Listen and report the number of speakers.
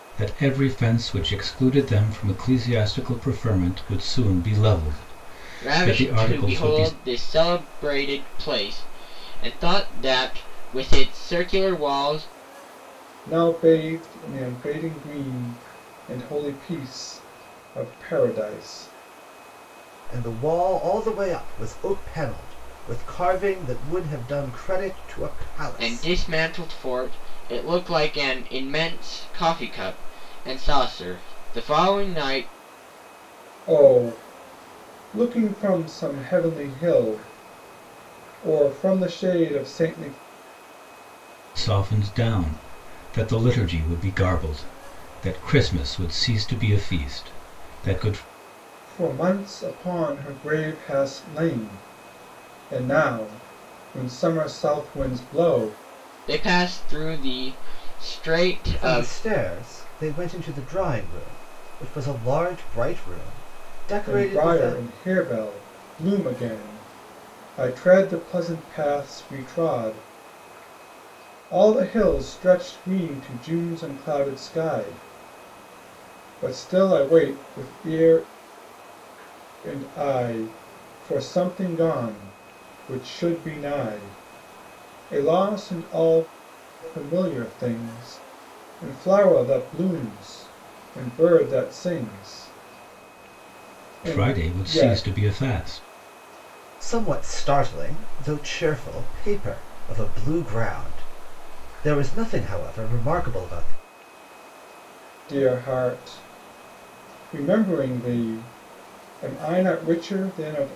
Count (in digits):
4